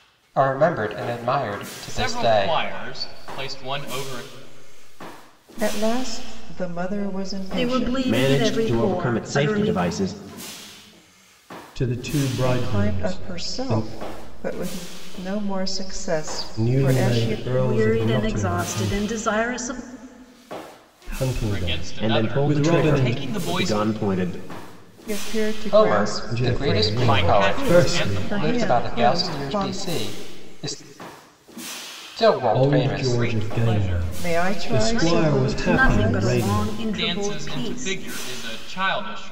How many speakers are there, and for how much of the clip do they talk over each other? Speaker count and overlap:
6, about 47%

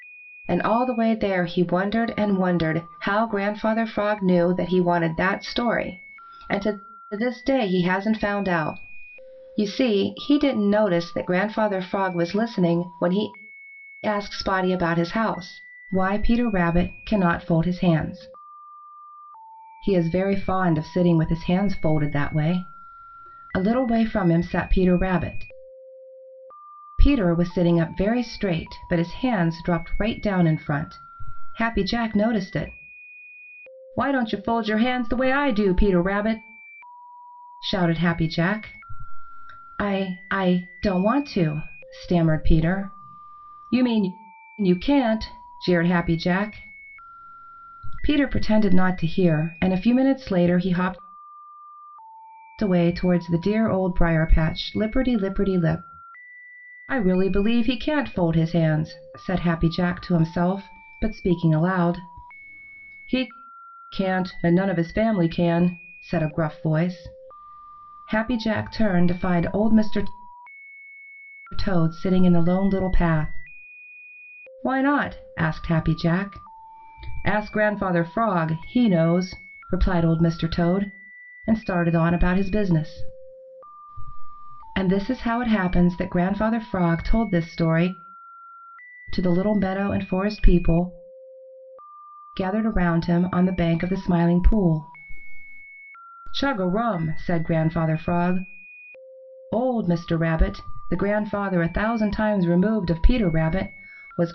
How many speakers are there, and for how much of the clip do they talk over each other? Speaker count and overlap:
1, no overlap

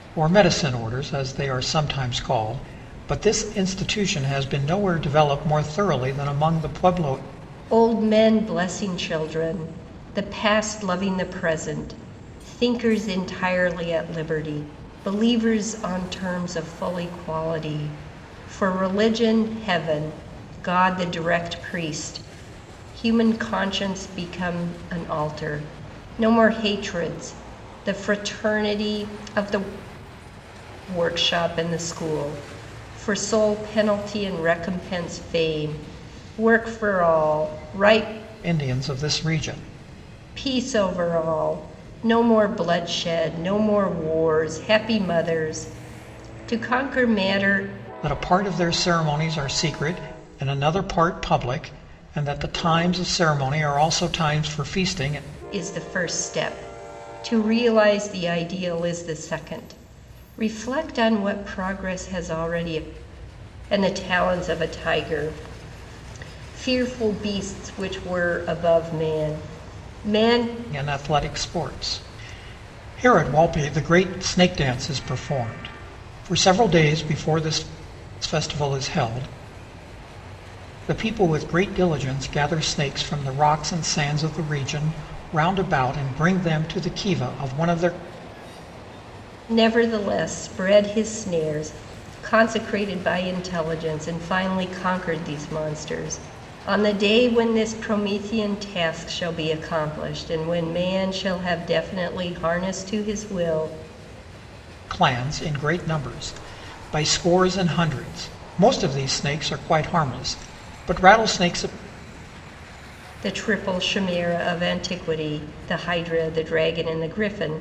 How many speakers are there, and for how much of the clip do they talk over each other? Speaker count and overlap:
2, no overlap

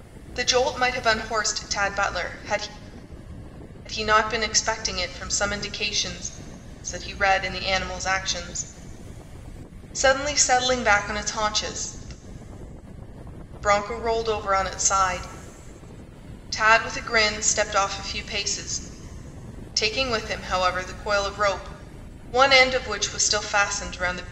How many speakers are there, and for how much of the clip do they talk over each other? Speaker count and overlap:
1, no overlap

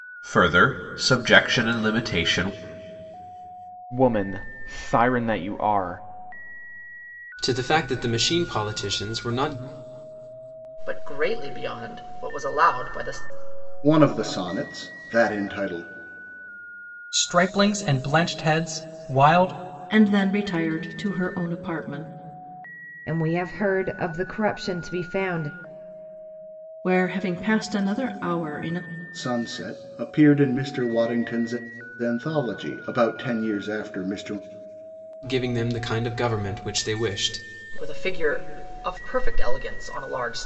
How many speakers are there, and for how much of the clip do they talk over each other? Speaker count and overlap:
8, no overlap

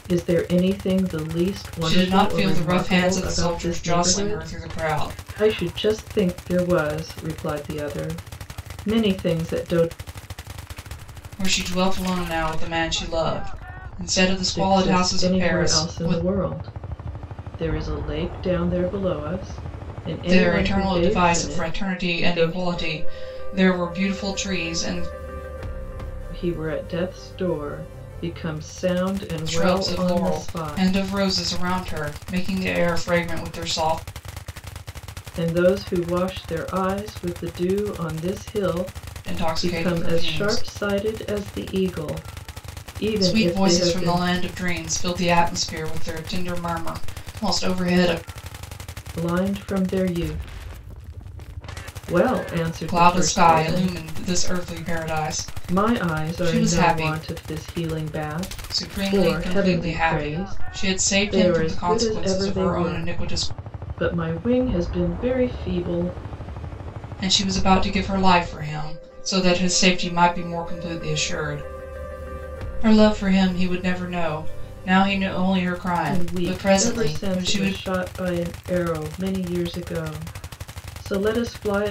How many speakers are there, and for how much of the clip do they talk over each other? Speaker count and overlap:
2, about 23%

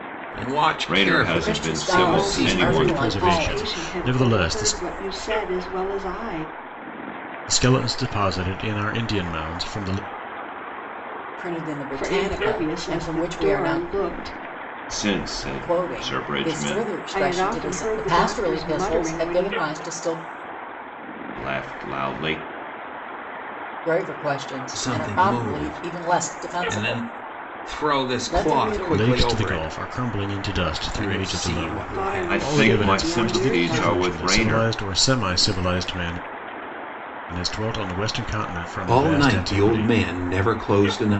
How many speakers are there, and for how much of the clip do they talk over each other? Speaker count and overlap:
5, about 46%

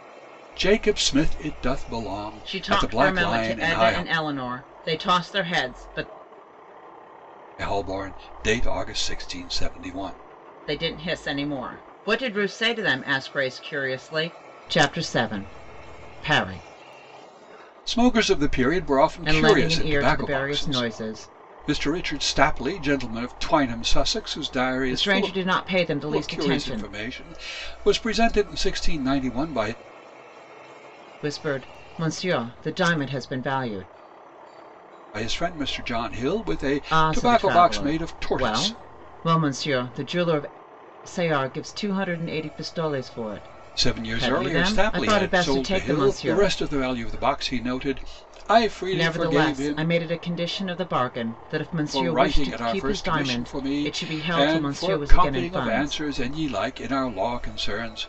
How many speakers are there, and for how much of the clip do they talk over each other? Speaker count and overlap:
2, about 25%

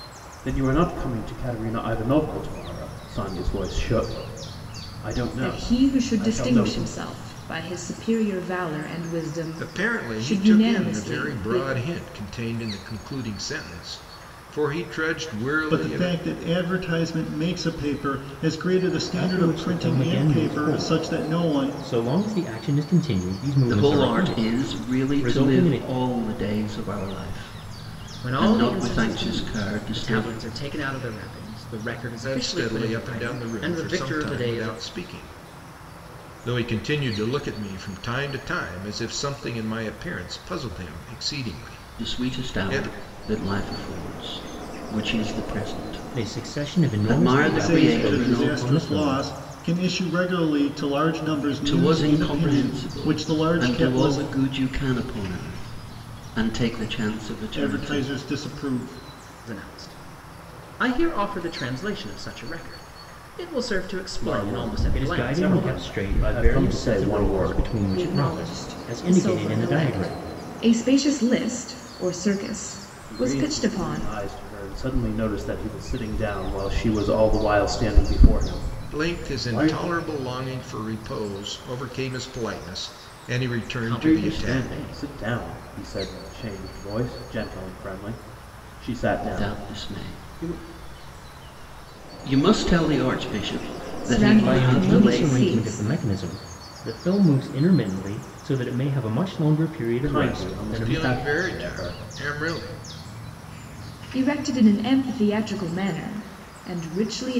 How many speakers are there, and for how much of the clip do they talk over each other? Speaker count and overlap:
7, about 33%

